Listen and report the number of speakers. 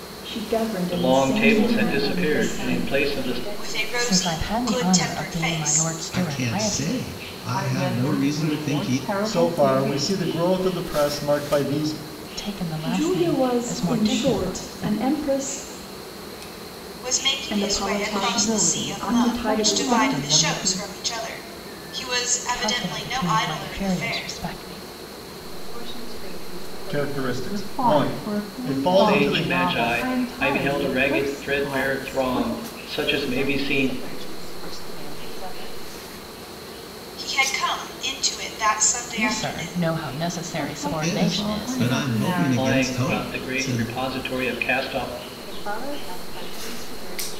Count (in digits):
8